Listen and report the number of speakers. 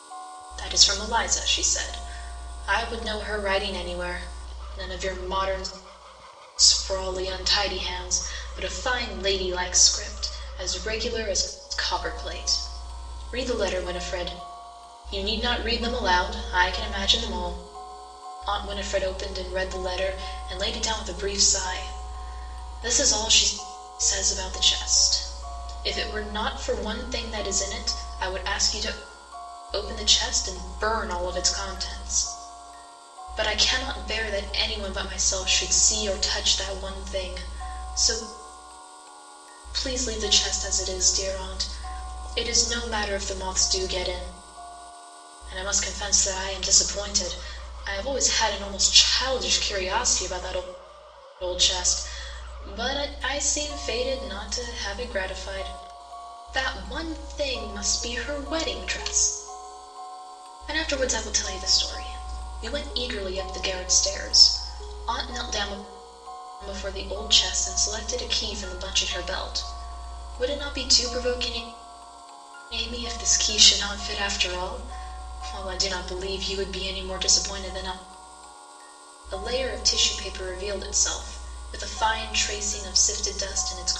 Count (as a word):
one